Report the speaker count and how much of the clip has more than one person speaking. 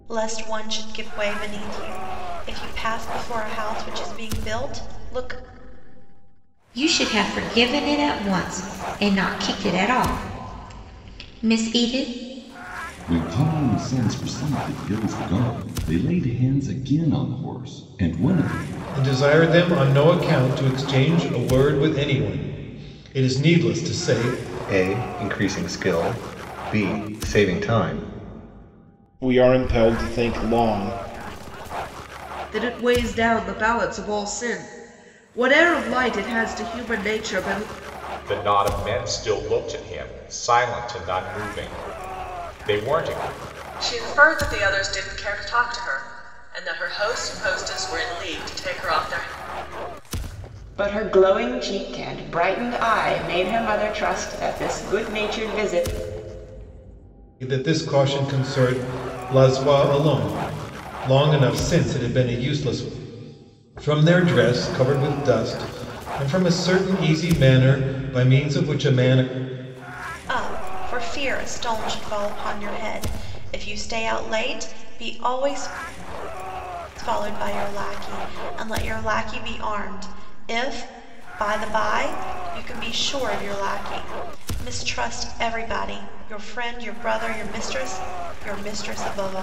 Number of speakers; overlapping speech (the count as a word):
ten, no overlap